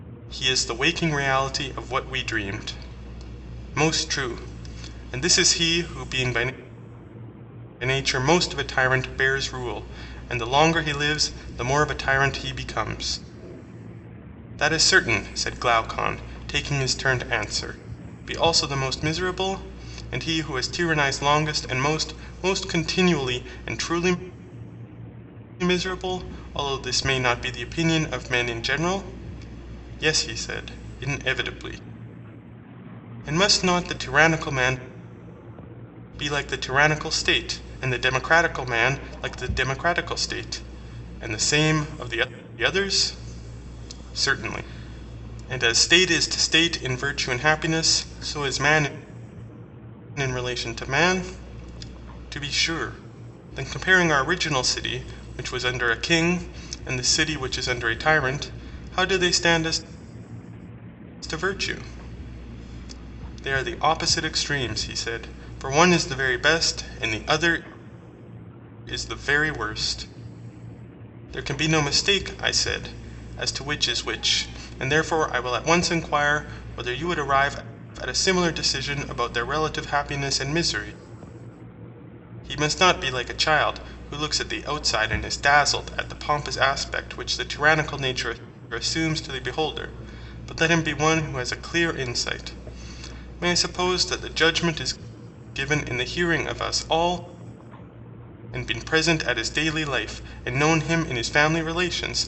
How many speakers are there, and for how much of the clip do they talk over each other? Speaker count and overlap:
1, no overlap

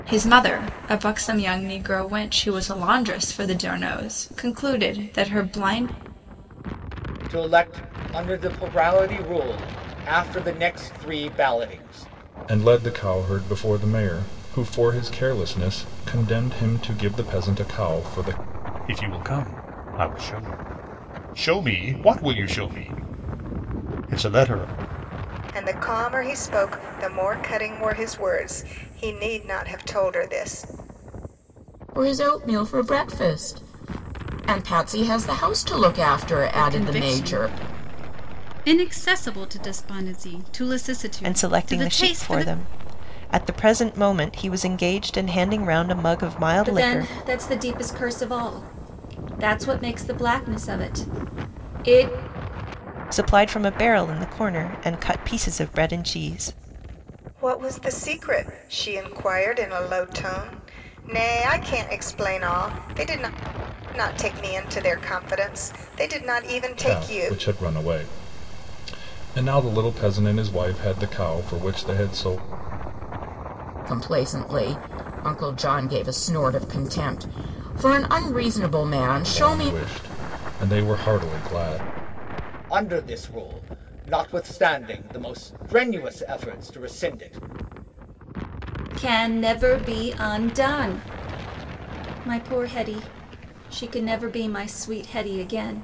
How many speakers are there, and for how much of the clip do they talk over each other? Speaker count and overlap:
9, about 4%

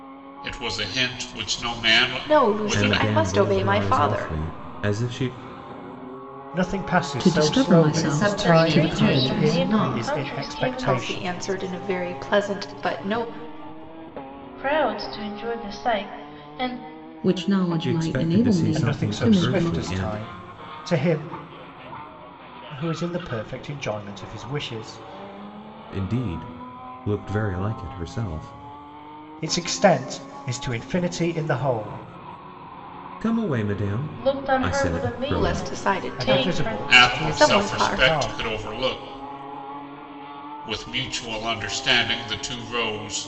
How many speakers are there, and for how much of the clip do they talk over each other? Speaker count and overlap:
7, about 30%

